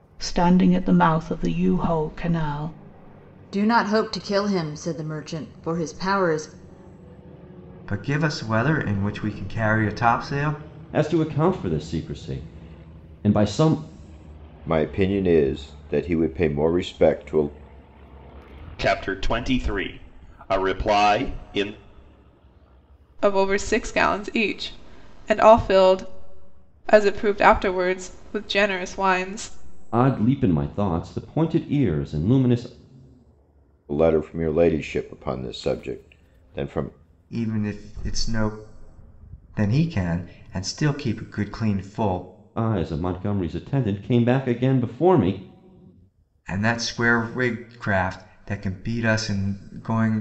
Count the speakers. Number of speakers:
seven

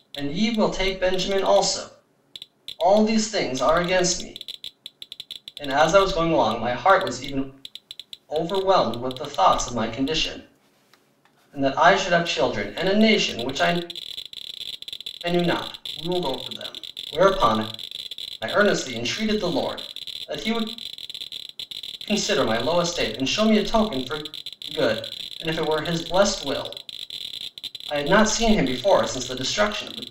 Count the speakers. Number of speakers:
one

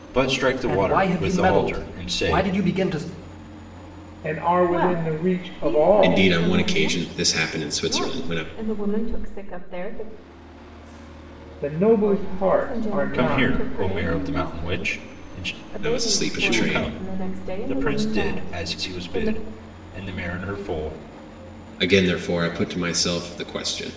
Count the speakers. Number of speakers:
five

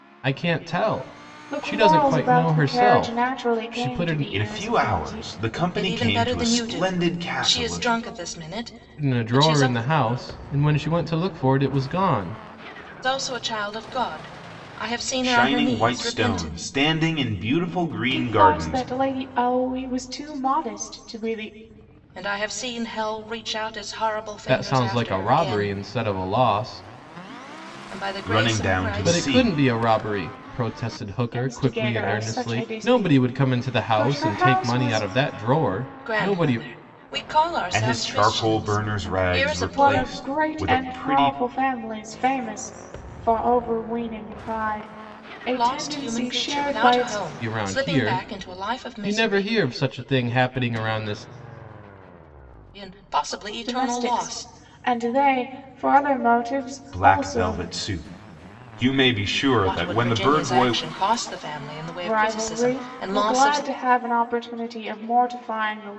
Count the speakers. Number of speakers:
four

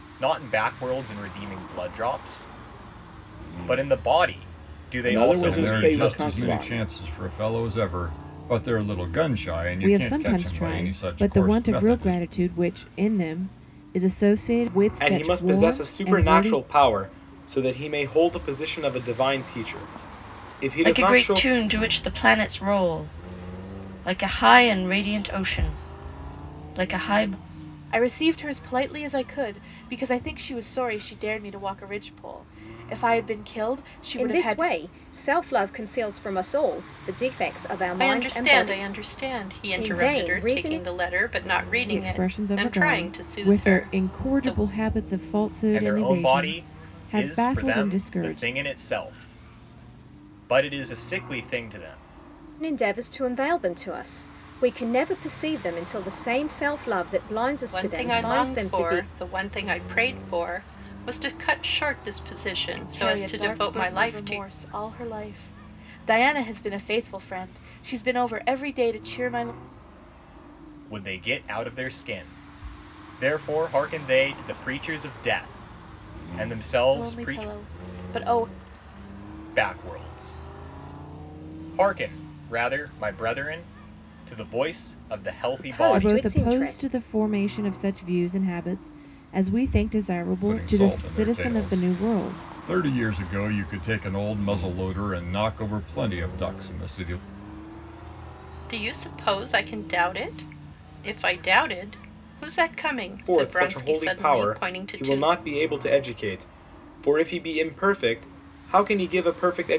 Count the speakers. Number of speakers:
nine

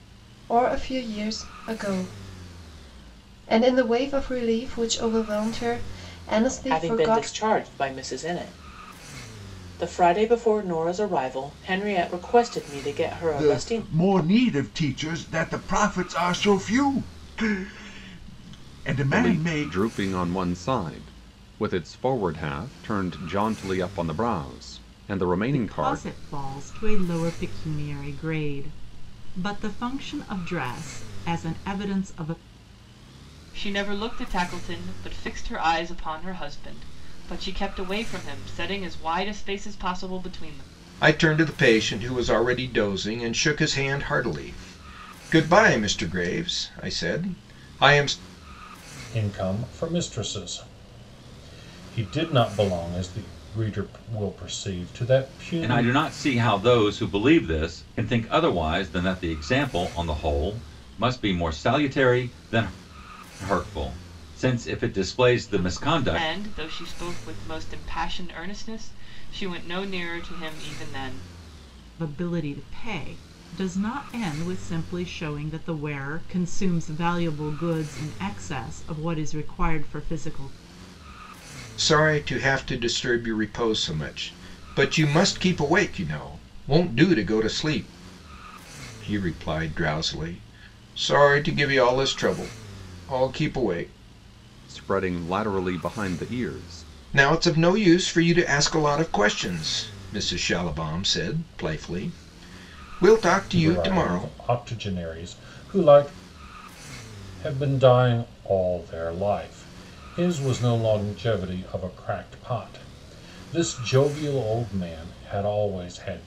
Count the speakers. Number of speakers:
nine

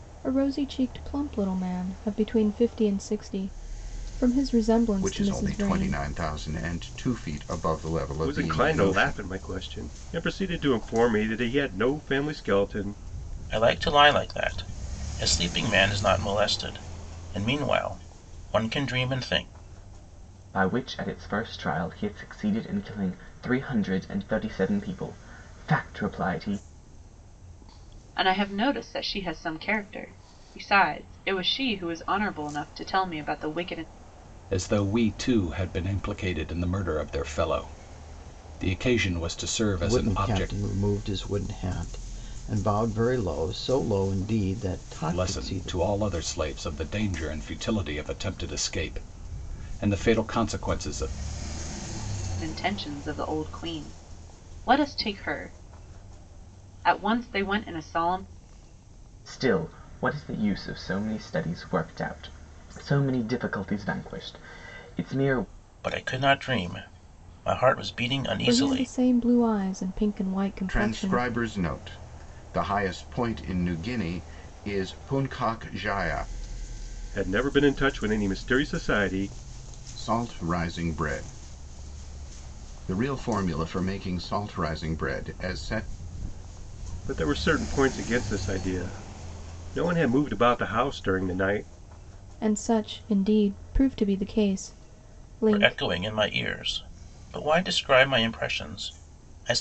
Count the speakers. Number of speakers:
eight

